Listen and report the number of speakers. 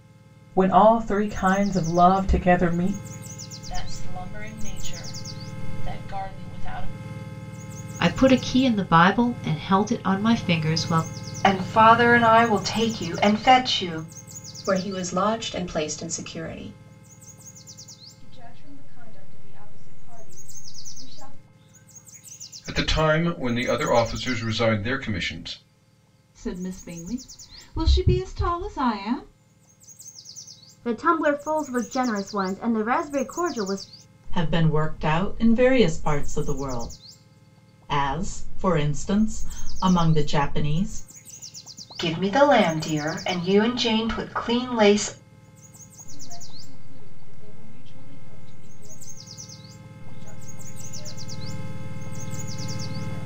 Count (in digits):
10